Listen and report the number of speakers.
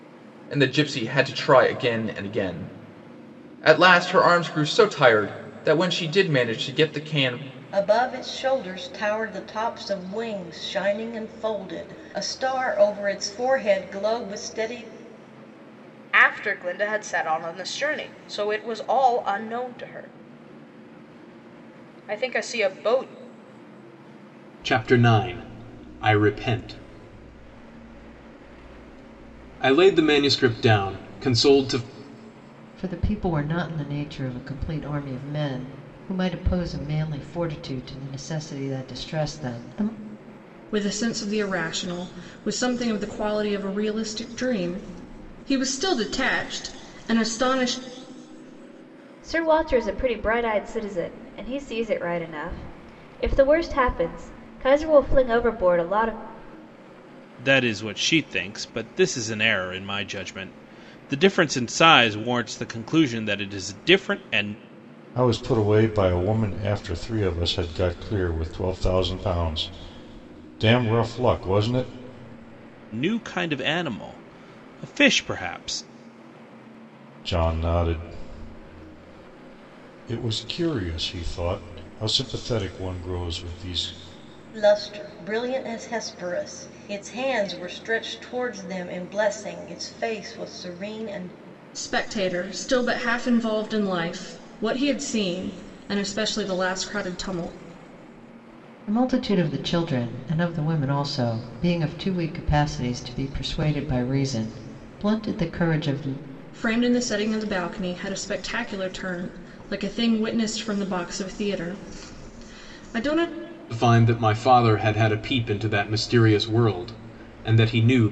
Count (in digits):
9